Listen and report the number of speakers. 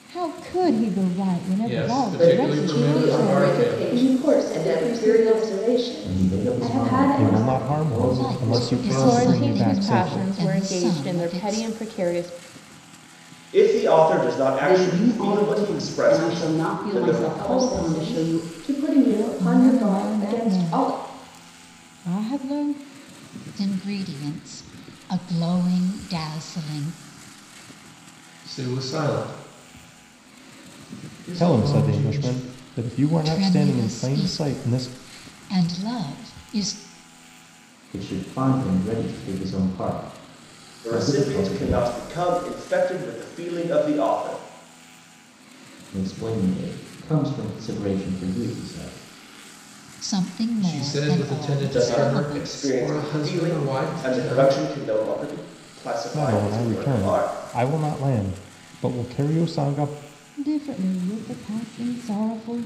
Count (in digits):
10